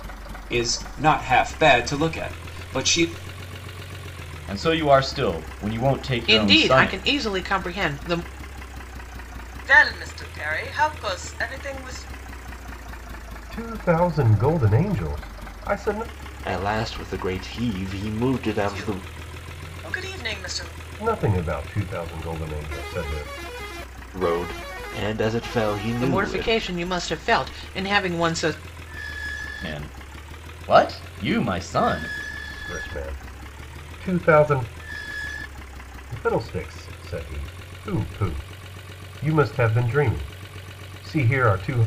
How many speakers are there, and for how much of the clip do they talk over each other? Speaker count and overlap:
6, about 4%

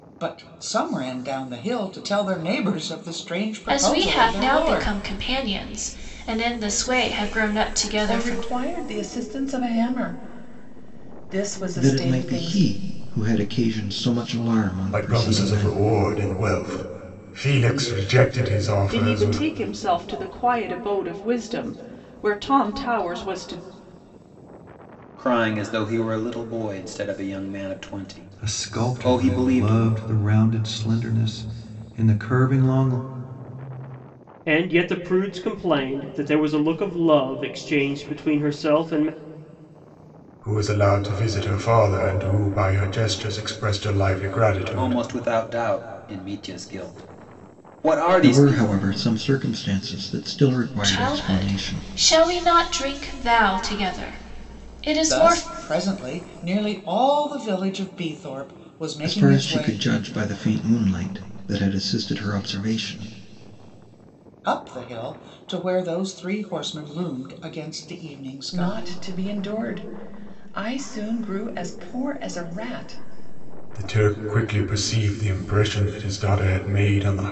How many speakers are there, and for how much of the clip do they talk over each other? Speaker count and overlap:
9, about 12%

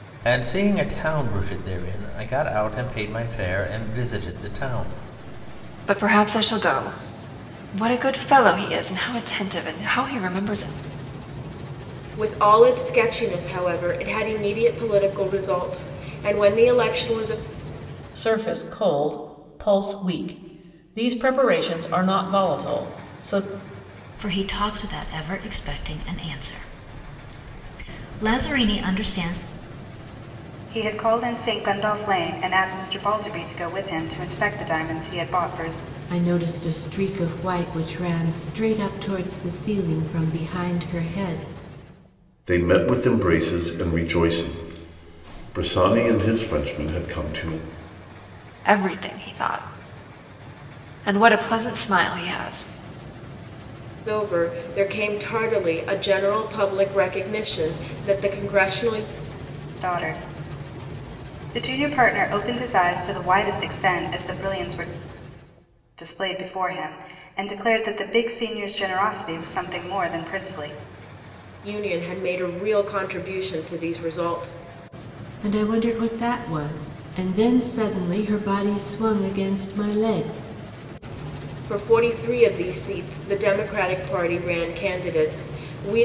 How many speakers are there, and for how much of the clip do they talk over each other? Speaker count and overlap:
8, no overlap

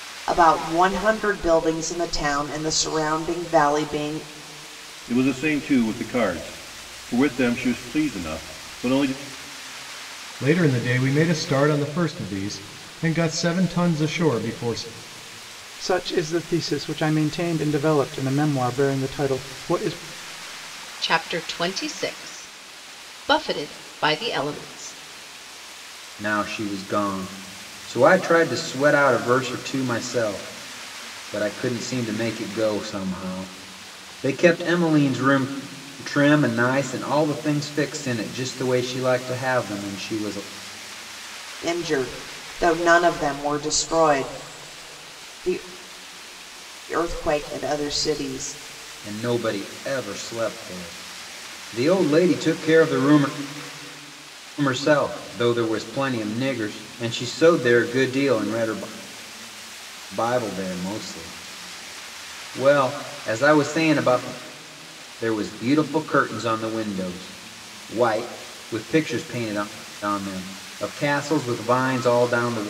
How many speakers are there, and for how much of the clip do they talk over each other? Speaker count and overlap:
6, no overlap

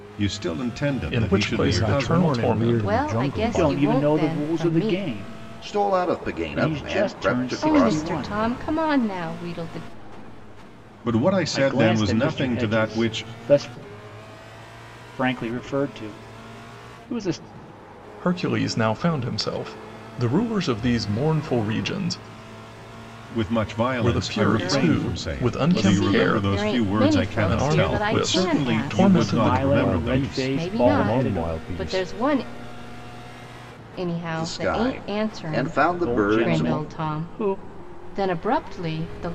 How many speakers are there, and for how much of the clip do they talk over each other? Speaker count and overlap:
6, about 48%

